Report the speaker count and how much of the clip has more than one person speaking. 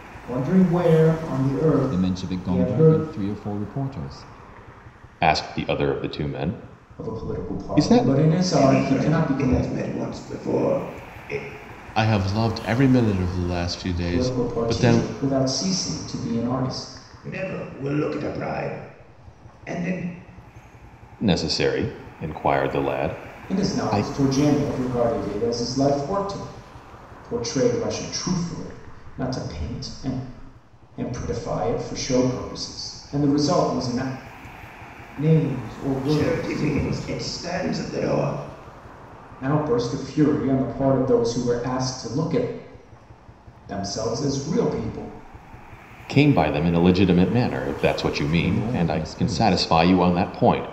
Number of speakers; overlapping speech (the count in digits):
6, about 16%